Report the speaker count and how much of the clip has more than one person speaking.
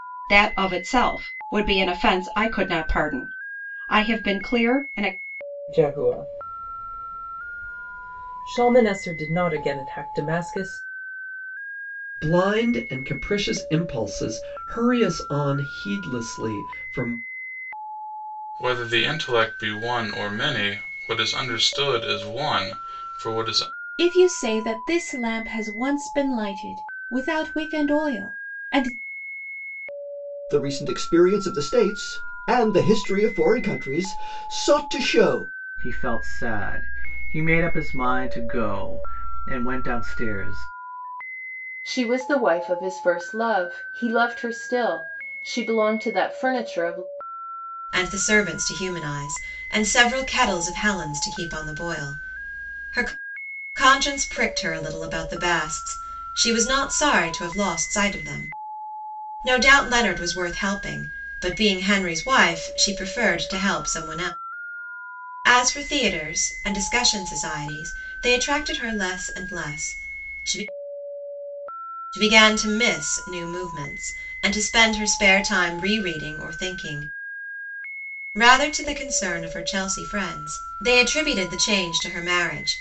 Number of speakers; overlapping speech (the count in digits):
9, no overlap